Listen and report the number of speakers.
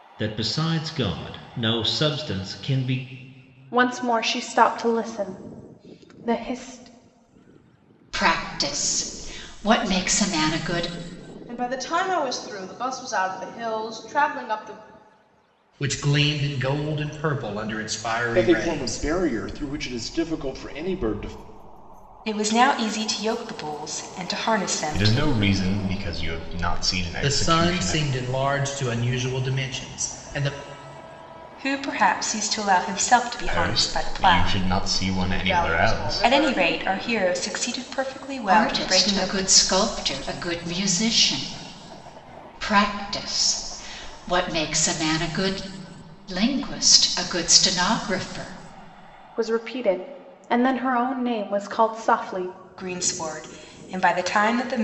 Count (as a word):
eight